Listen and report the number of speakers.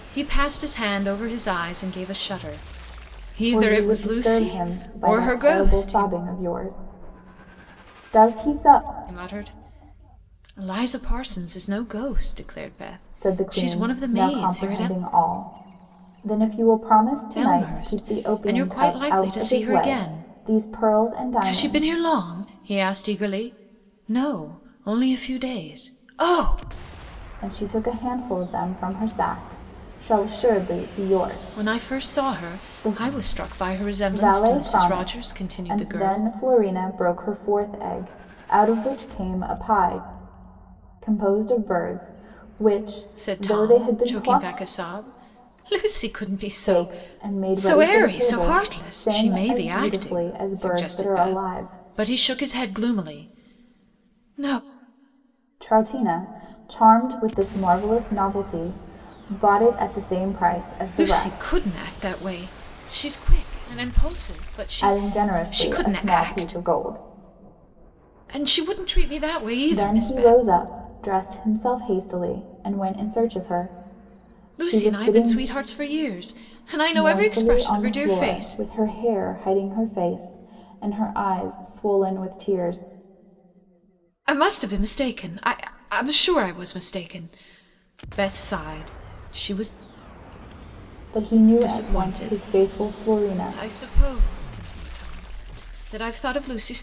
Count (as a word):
two